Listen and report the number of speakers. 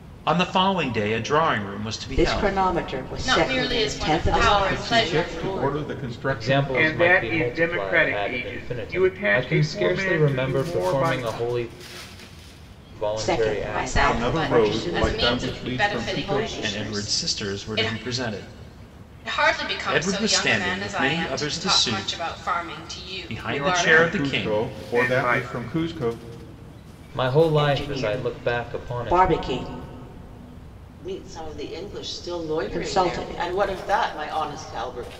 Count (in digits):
7